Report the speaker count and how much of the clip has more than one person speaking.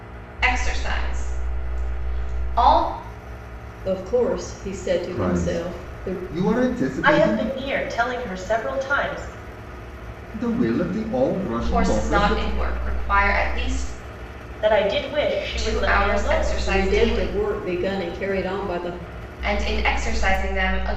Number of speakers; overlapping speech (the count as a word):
four, about 21%